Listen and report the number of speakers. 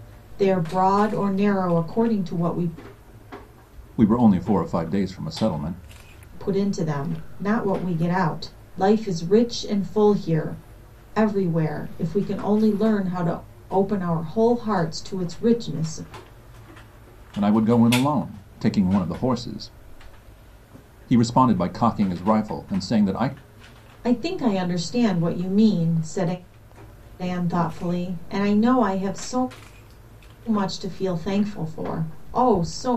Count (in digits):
2